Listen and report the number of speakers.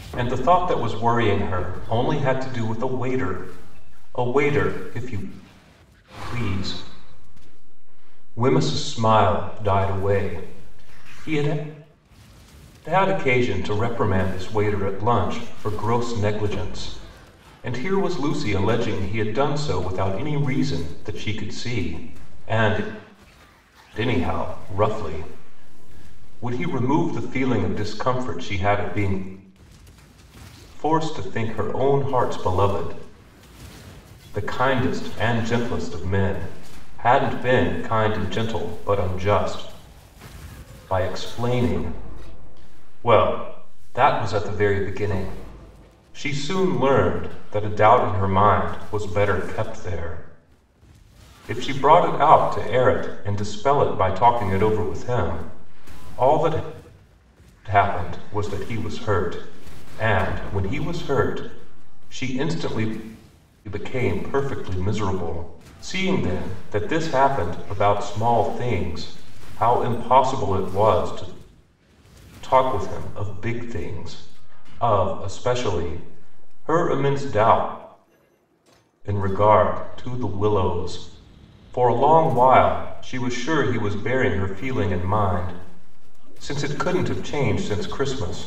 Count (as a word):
one